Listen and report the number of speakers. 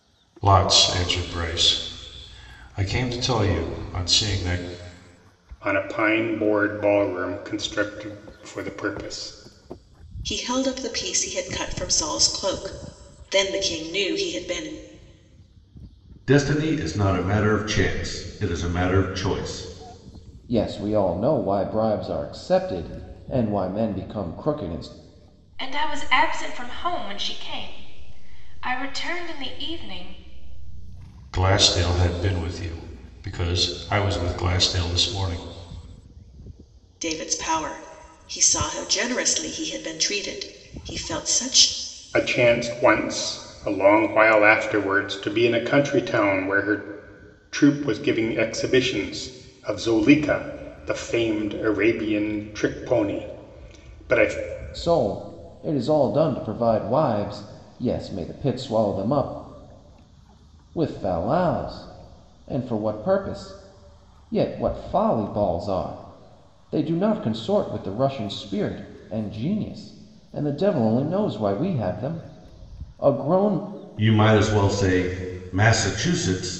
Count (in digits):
6